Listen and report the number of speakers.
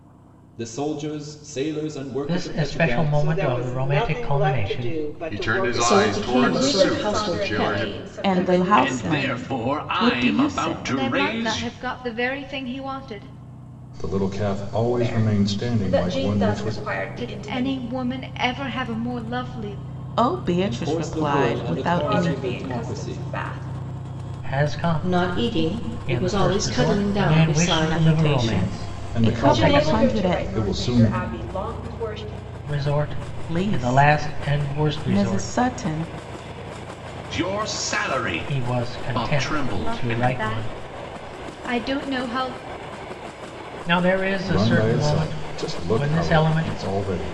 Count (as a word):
ten